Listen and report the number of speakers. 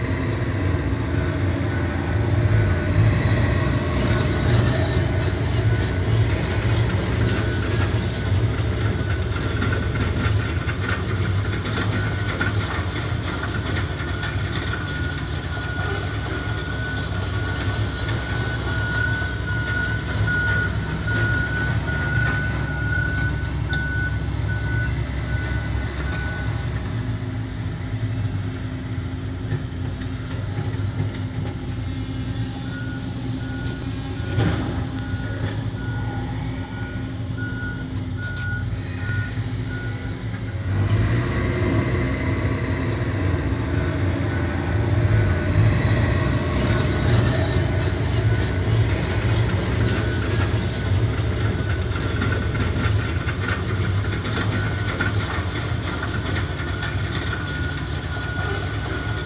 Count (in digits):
0